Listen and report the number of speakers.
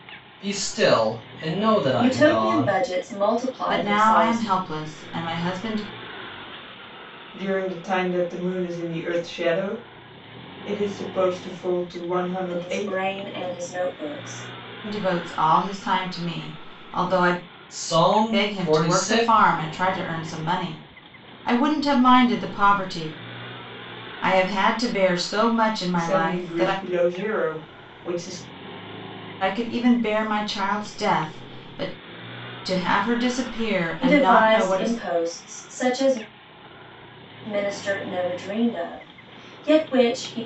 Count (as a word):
four